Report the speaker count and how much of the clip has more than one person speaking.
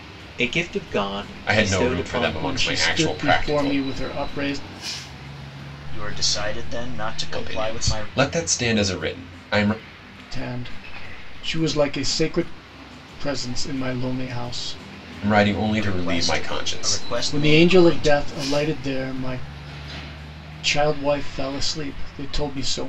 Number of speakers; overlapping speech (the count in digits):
4, about 23%